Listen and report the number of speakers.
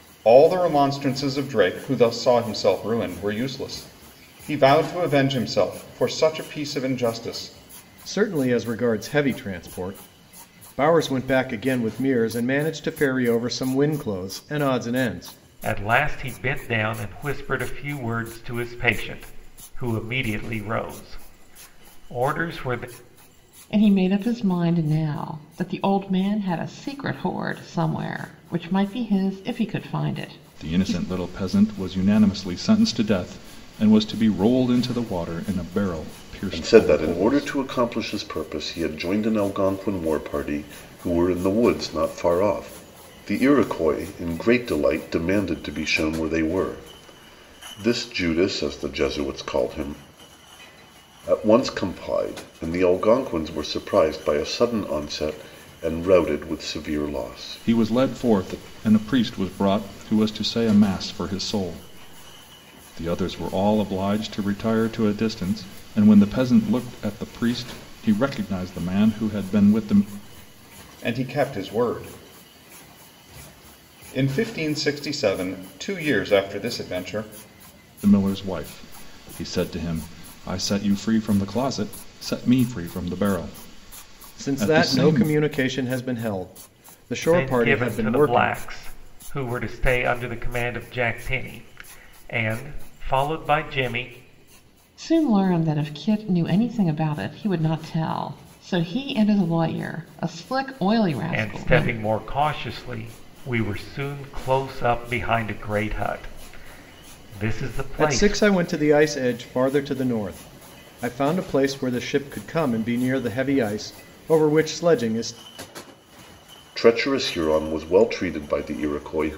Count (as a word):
six